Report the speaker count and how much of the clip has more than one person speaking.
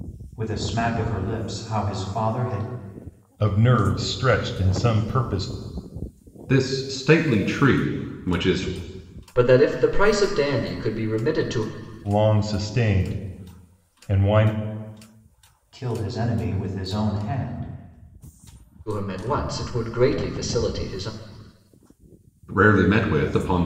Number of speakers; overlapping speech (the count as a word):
four, no overlap